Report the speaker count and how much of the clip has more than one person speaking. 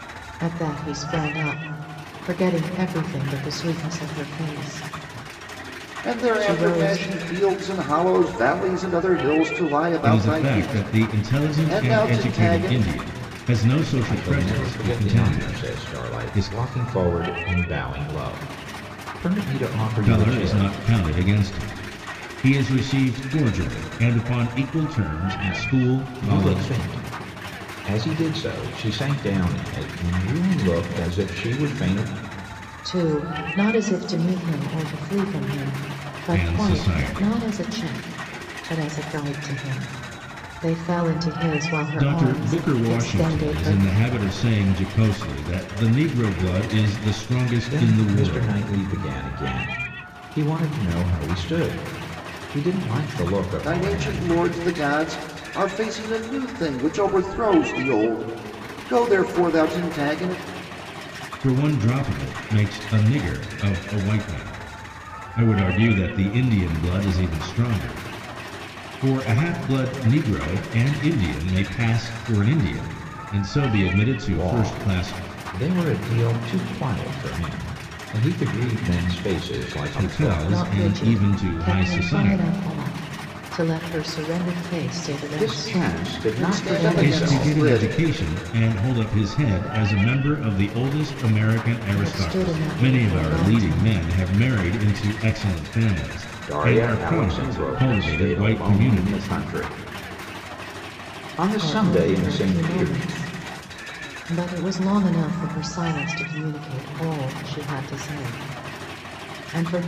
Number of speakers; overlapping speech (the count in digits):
4, about 24%